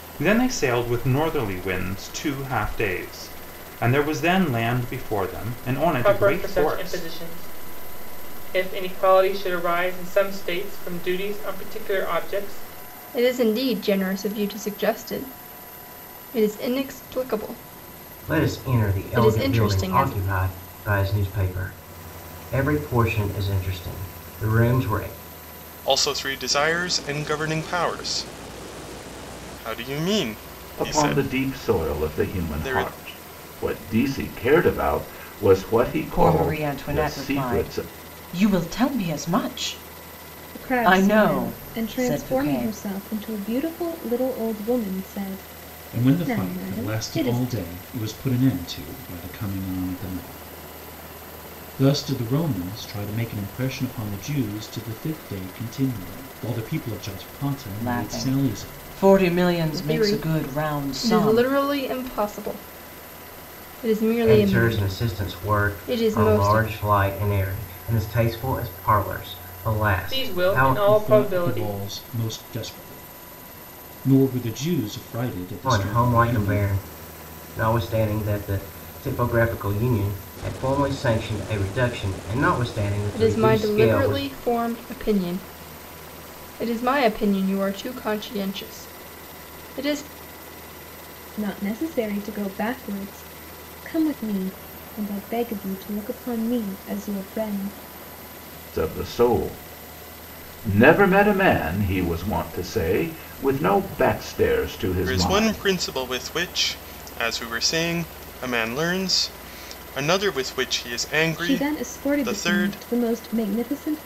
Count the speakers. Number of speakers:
9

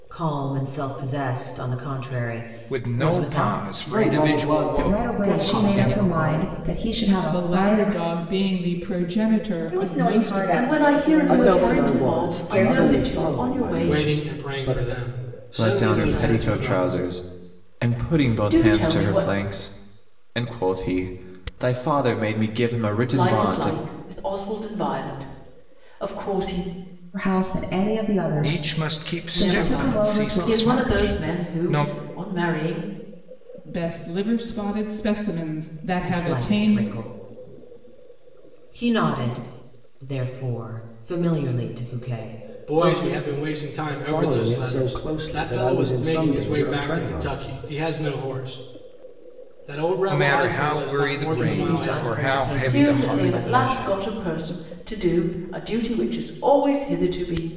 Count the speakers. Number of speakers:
10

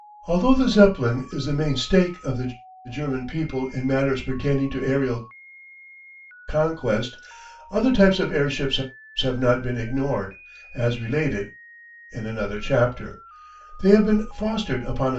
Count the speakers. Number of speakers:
1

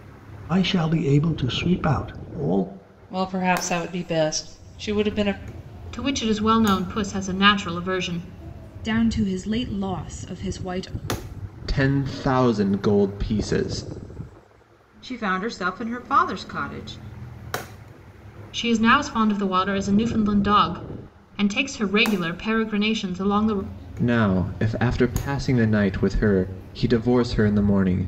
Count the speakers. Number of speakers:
6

